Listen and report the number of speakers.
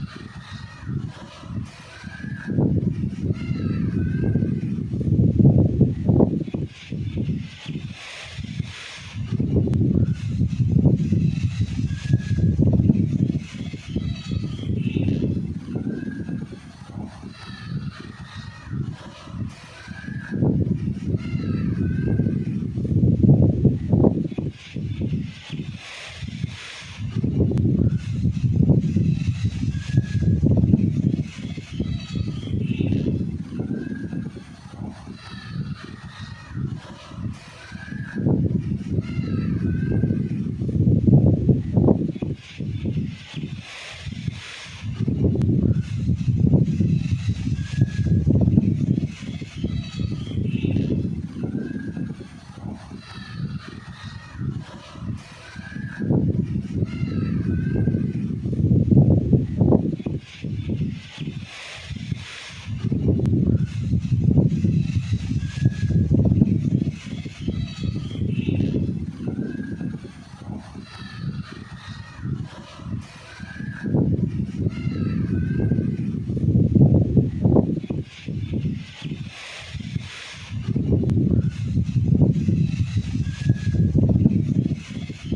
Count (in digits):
0